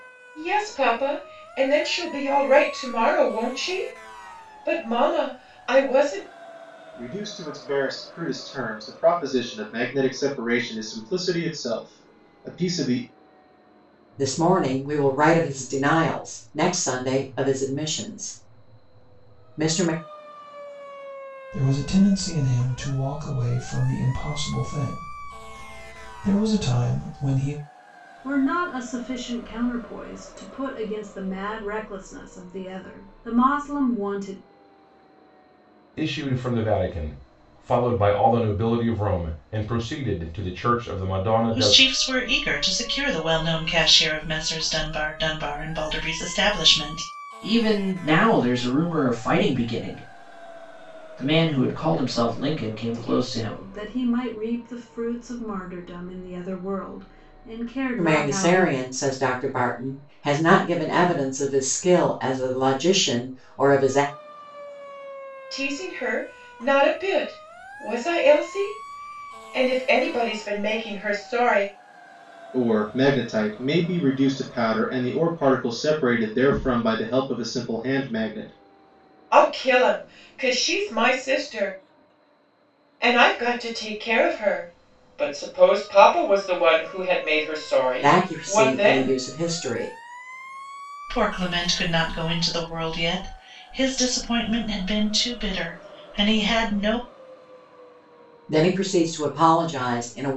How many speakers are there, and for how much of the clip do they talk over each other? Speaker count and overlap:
eight, about 3%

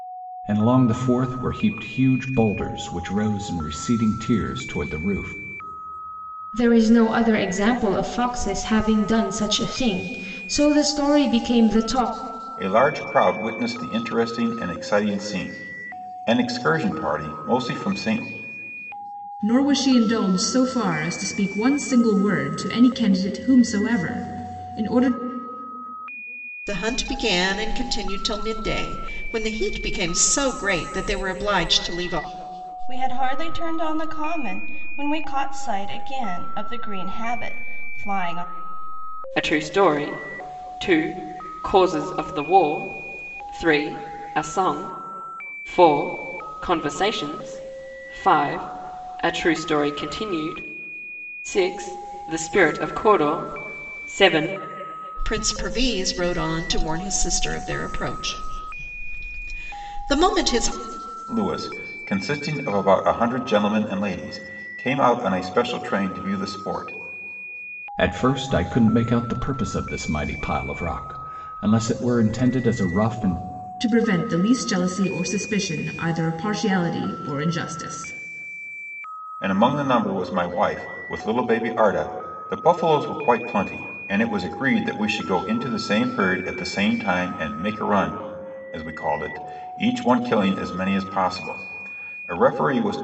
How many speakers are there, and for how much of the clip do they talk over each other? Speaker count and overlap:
seven, no overlap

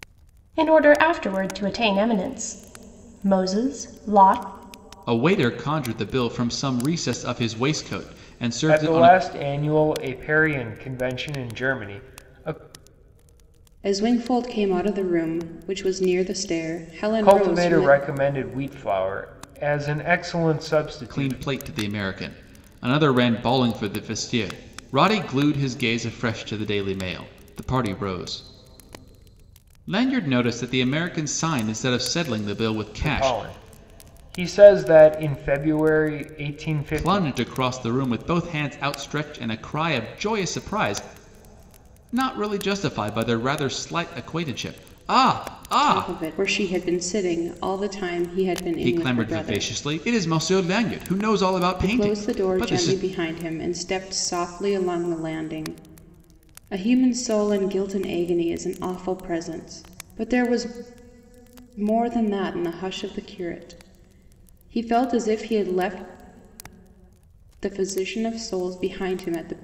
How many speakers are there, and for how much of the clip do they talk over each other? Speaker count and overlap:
four, about 8%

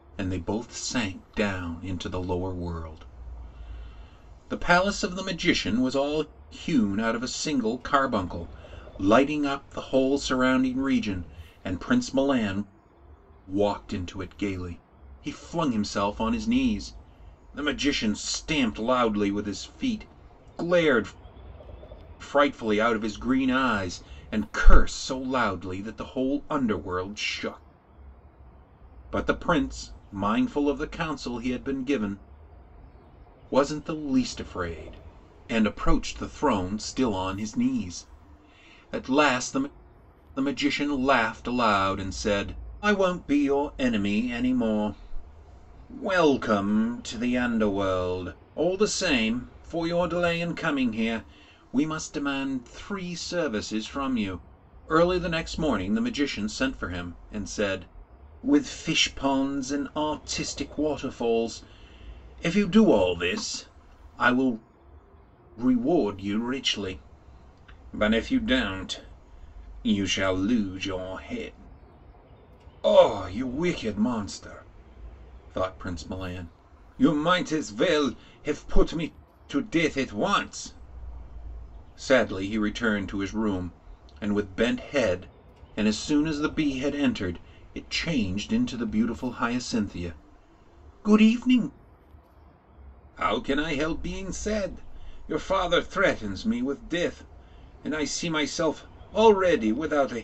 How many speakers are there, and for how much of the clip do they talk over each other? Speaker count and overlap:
one, no overlap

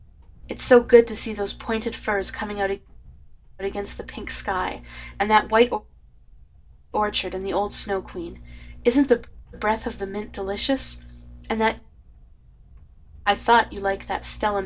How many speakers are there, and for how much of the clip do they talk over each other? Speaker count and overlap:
one, no overlap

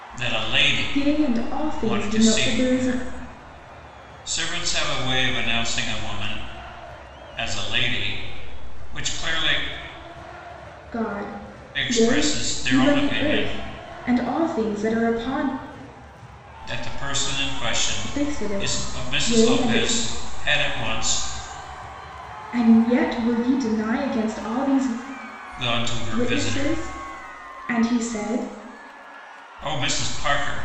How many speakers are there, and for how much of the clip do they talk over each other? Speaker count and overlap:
two, about 21%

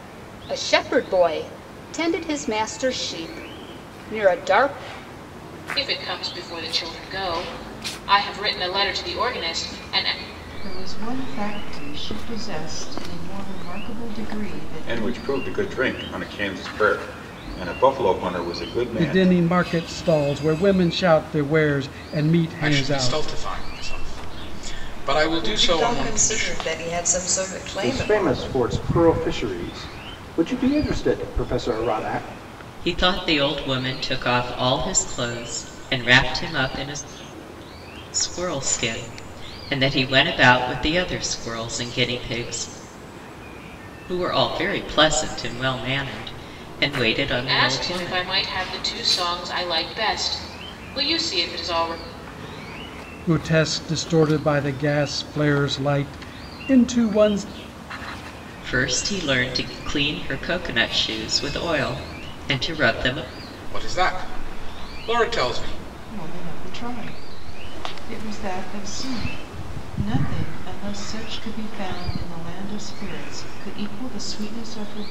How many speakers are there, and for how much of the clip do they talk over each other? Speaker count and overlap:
nine, about 6%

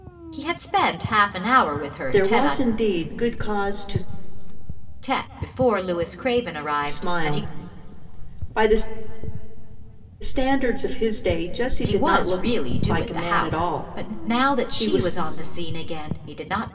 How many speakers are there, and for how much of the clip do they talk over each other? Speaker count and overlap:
two, about 25%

